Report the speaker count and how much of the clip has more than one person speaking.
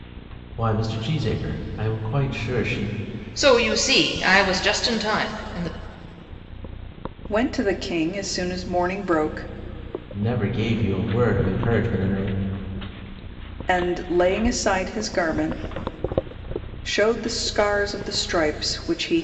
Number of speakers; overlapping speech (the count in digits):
3, no overlap